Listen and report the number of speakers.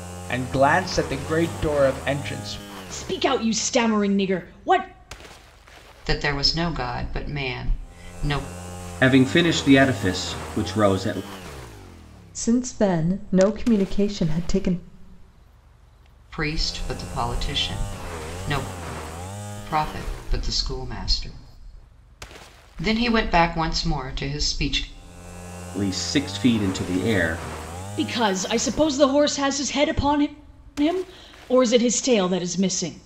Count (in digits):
5